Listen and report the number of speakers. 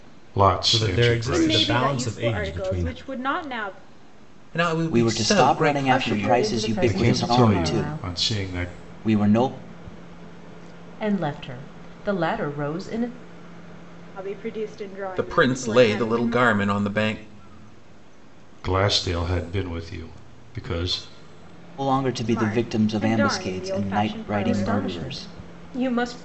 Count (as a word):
six